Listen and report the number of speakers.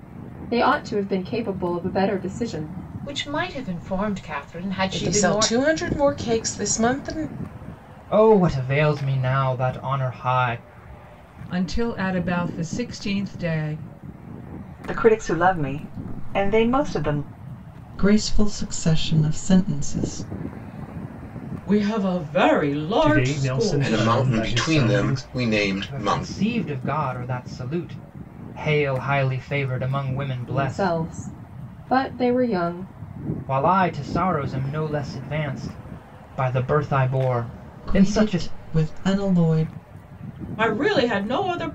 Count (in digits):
10